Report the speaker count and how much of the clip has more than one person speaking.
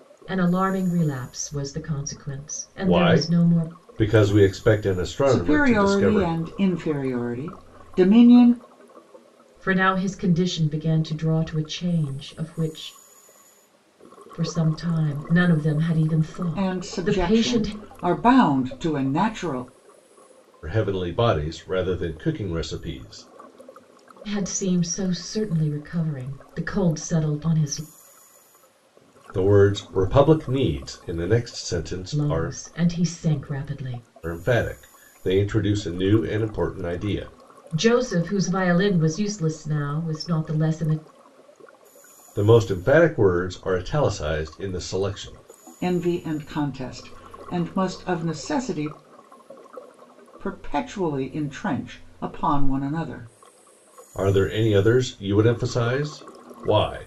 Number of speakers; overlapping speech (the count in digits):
3, about 6%